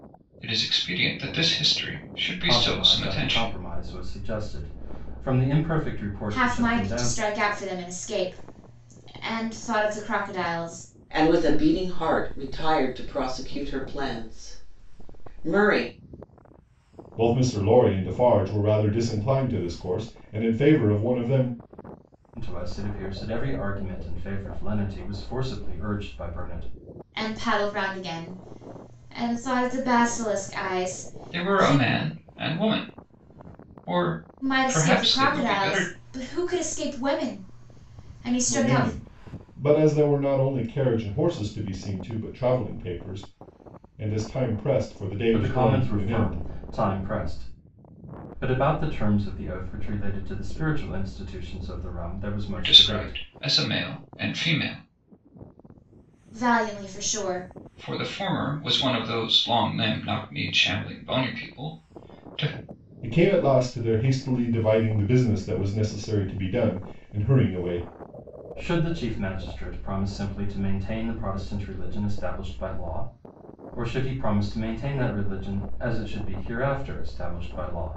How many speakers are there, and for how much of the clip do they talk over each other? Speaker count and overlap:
5, about 8%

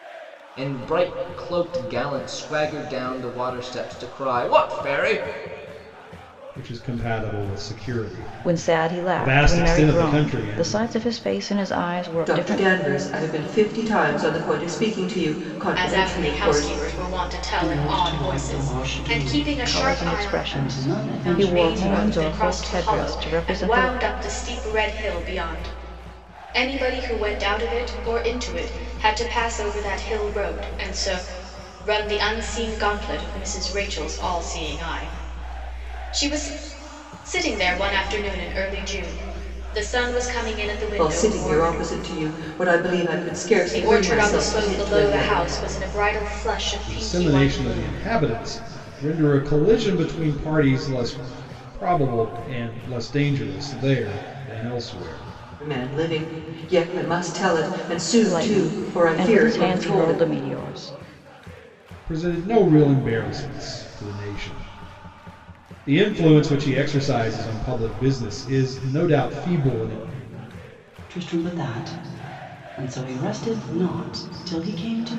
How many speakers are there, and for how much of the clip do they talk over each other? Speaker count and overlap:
6, about 22%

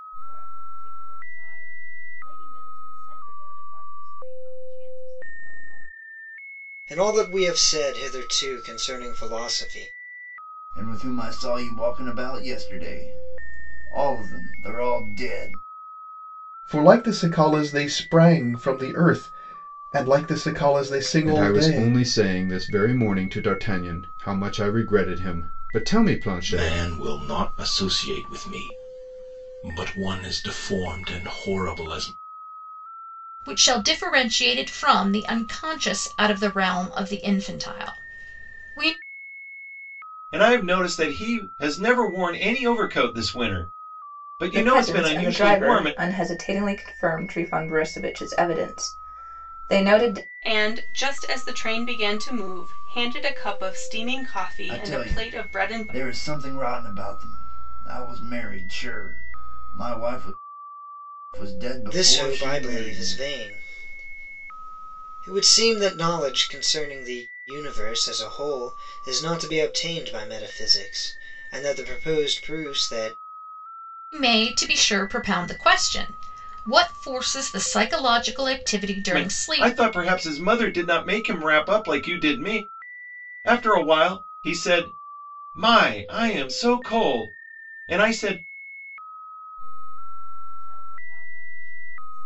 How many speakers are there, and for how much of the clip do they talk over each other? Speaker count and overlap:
10, about 6%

